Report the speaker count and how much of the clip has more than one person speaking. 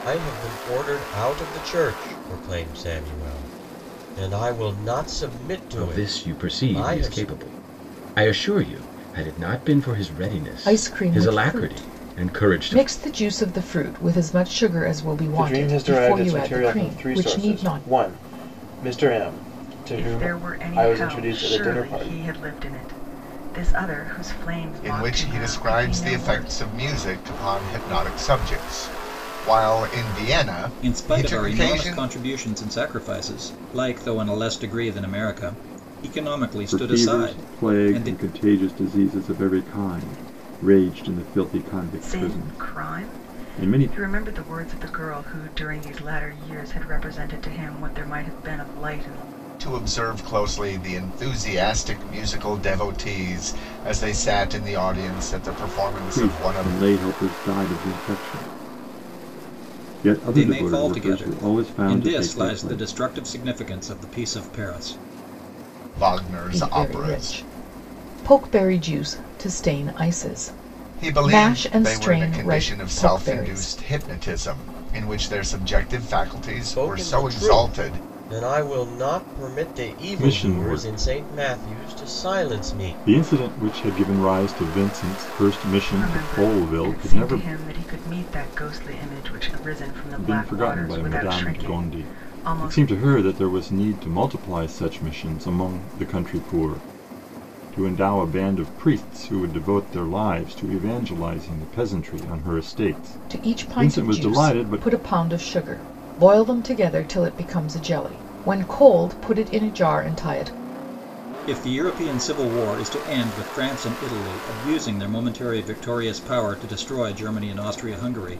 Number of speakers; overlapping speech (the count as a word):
eight, about 28%